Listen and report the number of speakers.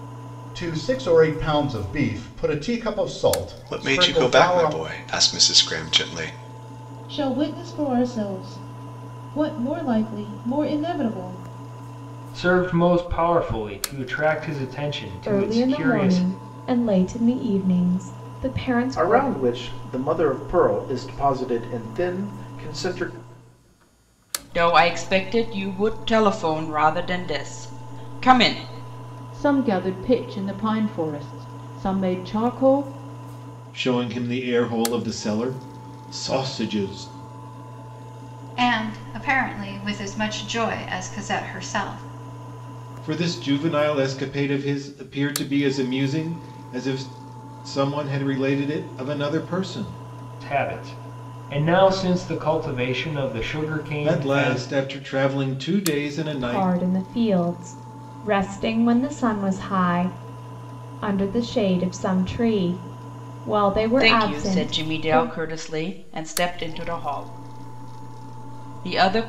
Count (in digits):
10